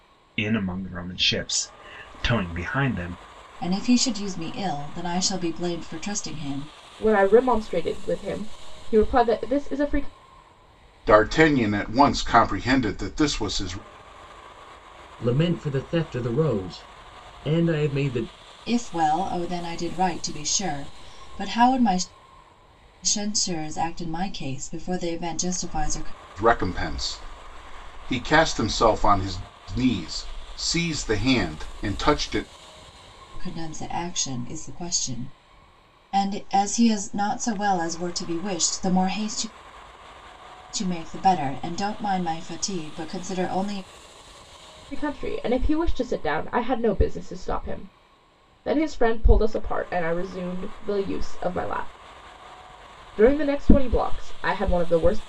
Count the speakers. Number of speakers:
5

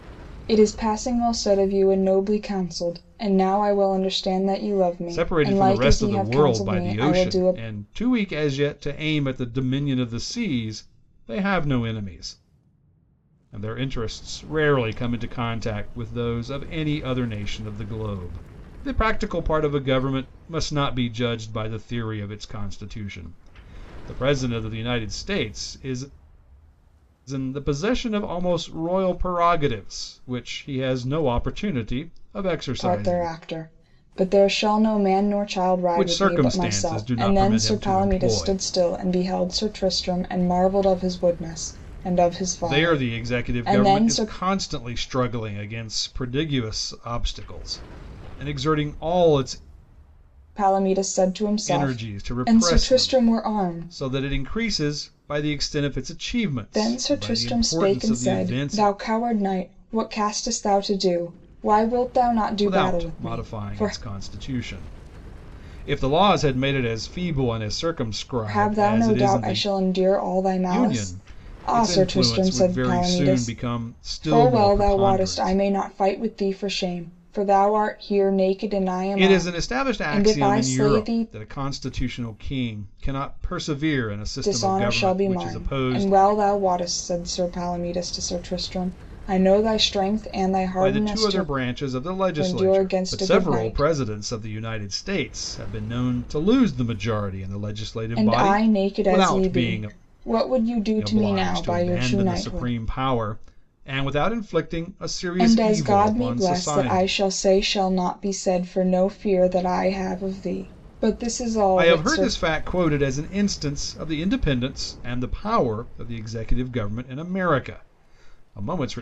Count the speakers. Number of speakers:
2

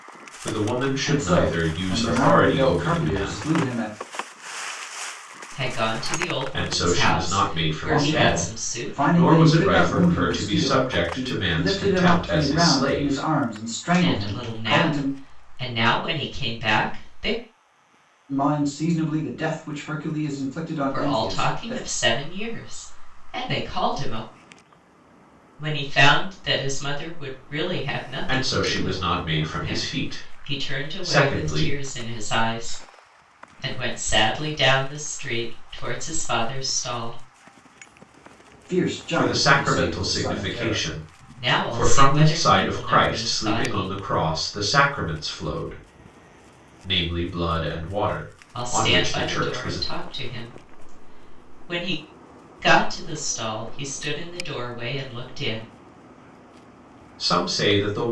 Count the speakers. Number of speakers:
3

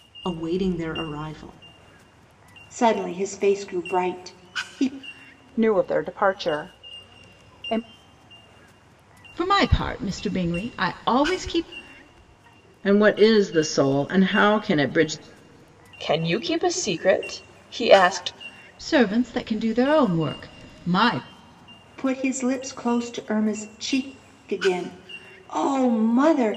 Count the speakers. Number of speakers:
6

